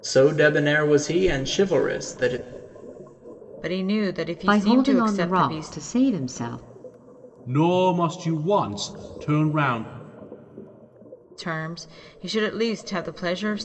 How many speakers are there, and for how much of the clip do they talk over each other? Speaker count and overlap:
4, about 11%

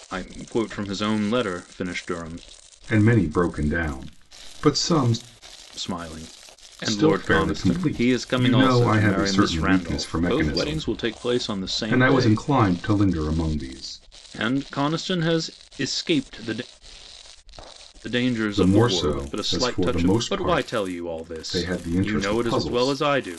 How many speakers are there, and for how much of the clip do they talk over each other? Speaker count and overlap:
2, about 35%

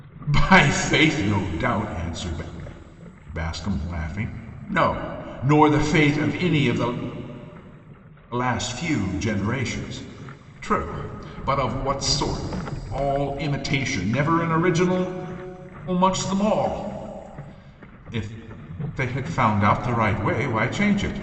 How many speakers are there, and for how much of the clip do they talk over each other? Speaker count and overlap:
1, no overlap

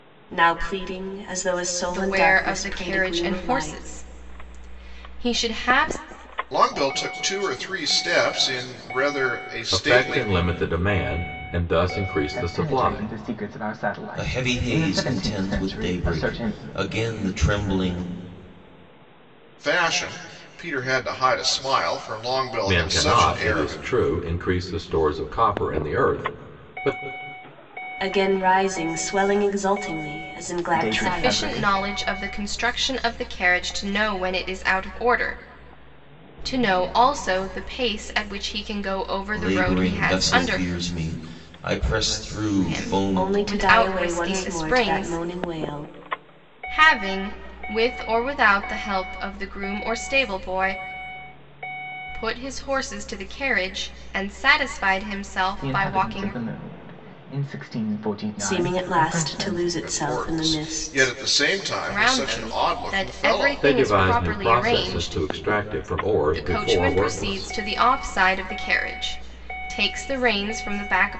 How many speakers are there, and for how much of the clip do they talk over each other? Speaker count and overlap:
6, about 28%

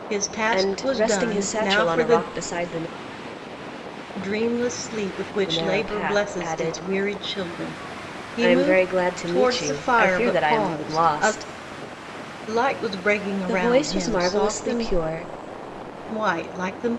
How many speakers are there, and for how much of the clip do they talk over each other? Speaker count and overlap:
2, about 42%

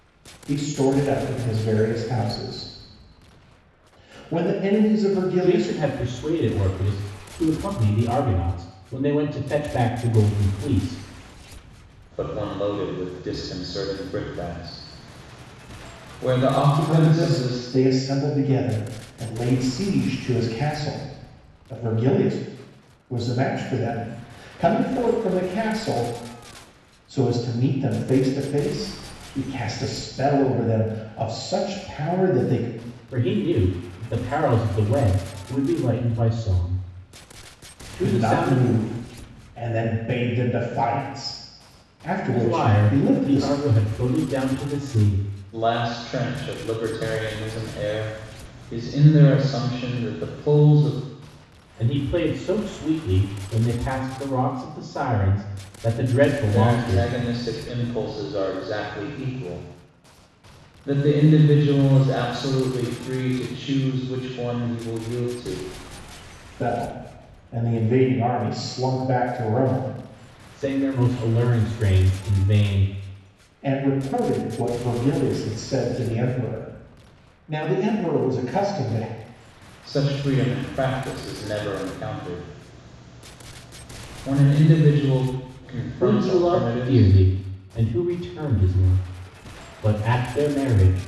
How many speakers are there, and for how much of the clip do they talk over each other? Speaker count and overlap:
3, about 6%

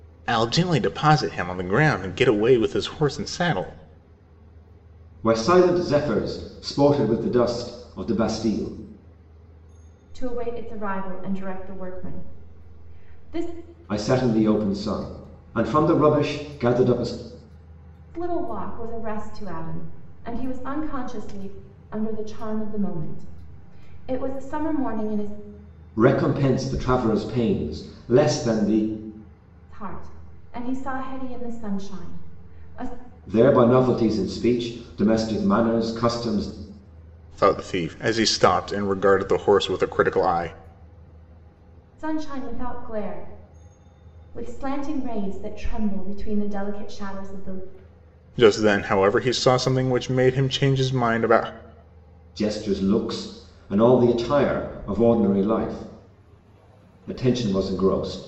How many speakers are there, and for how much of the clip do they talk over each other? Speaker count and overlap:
3, no overlap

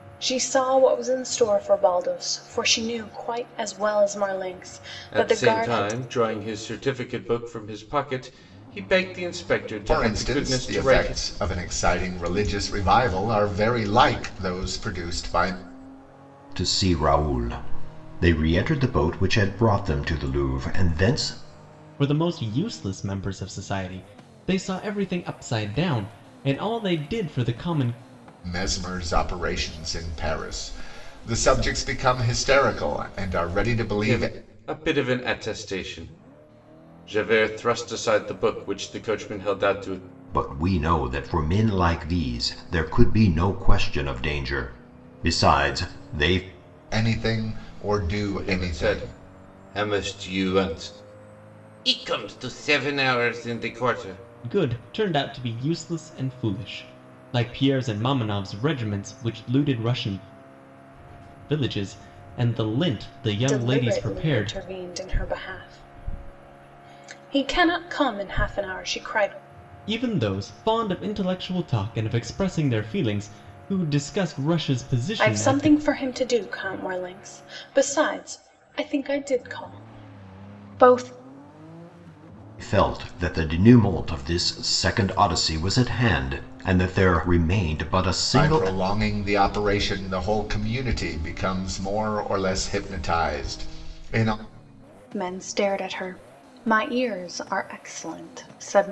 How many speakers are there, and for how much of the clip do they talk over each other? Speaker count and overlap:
5, about 6%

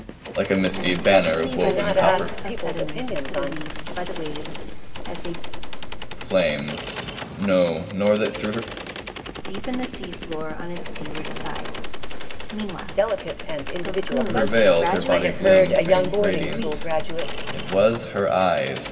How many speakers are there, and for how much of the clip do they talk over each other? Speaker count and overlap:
3, about 39%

